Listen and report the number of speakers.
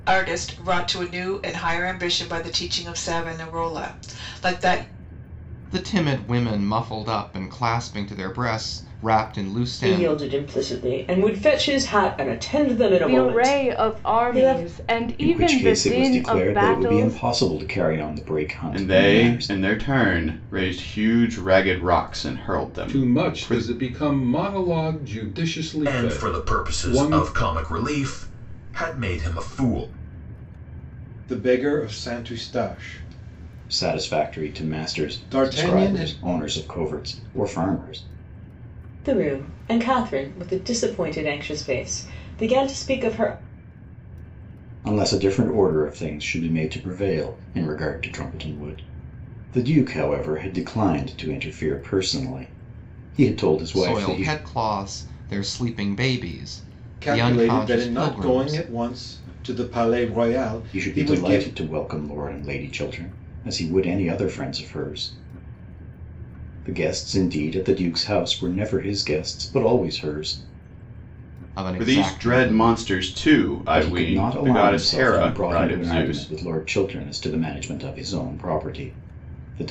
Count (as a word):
nine